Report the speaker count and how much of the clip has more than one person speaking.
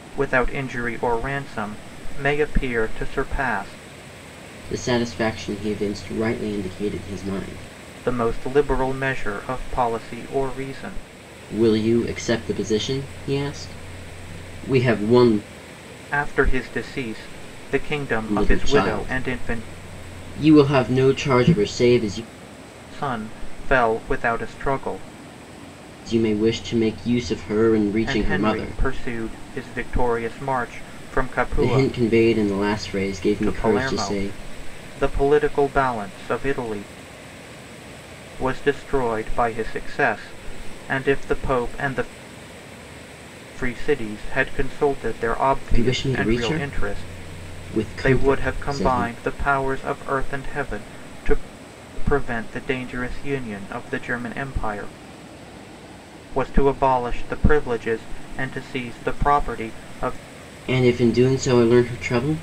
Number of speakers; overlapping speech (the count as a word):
two, about 10%